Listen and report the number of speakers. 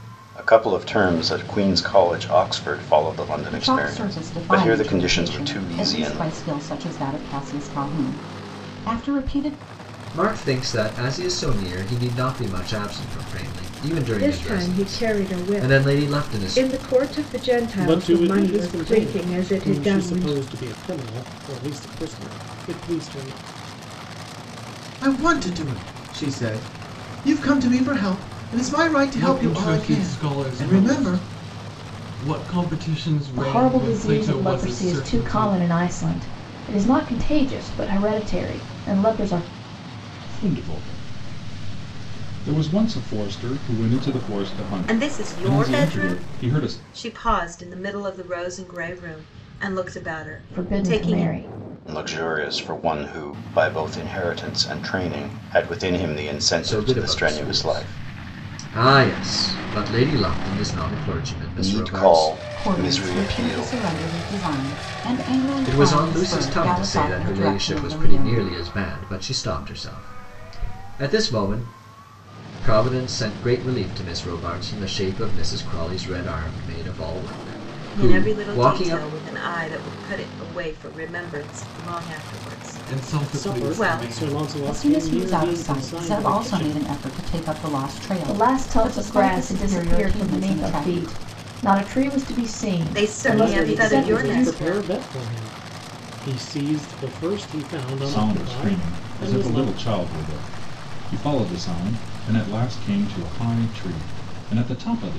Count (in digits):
10